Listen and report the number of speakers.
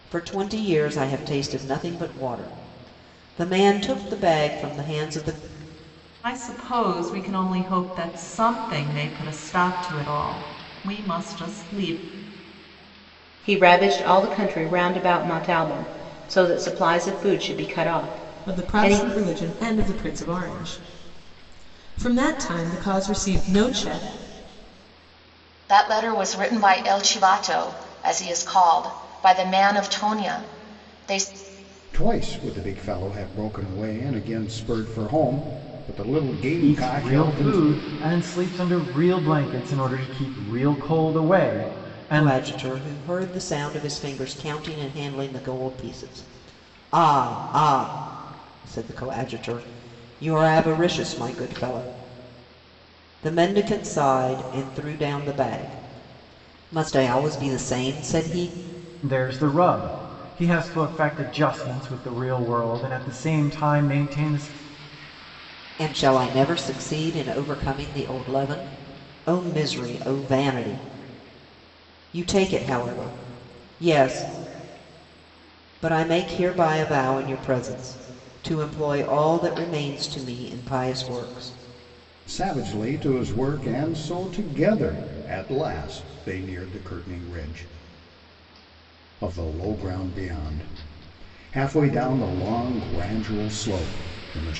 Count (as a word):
seven